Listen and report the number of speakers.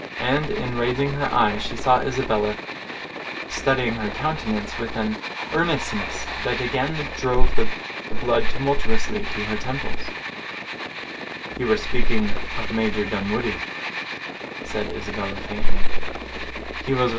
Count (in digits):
1